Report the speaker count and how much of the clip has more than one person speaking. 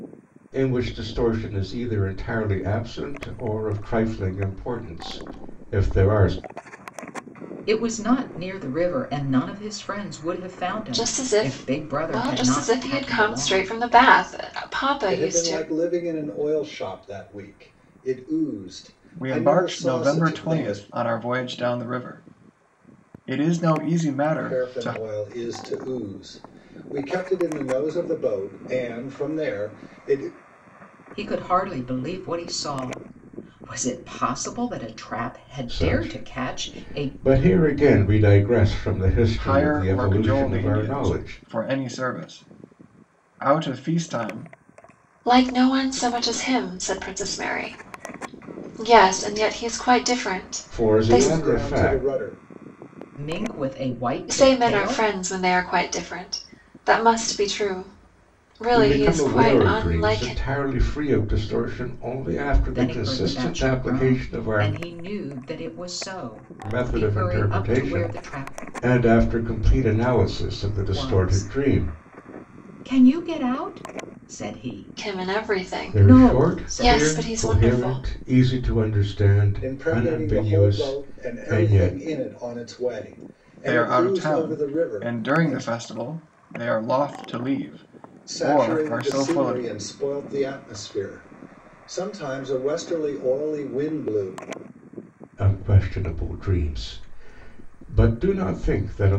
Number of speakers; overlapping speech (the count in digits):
5, about 28%